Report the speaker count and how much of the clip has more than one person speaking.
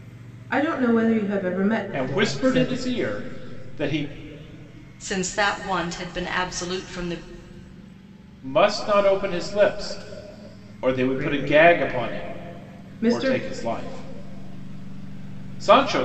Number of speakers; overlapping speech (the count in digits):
3, about 16%